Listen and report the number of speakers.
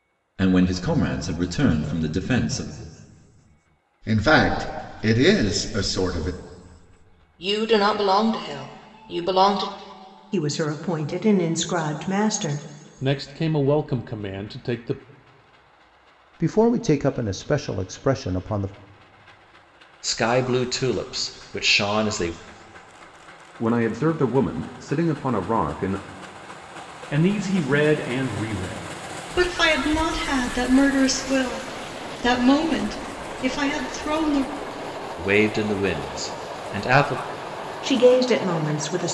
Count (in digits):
10